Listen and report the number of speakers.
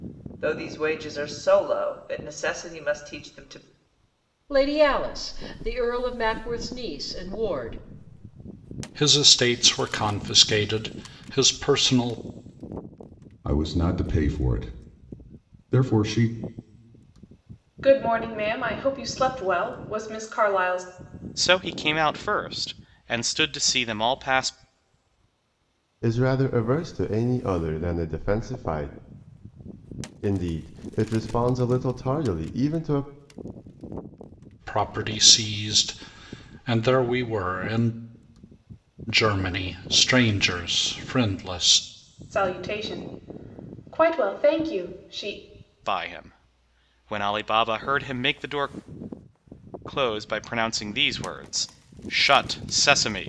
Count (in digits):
7